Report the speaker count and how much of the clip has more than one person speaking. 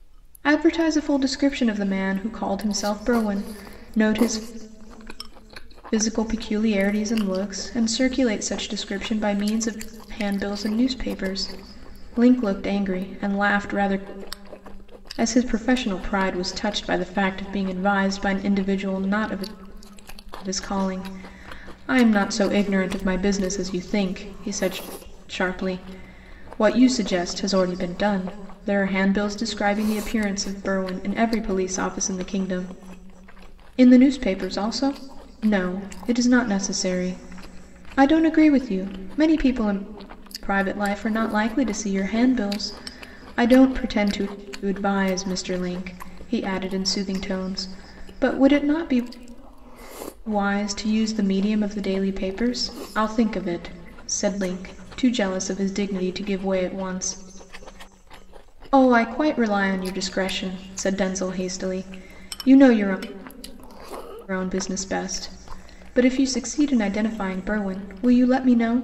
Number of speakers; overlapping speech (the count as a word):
one, no overlap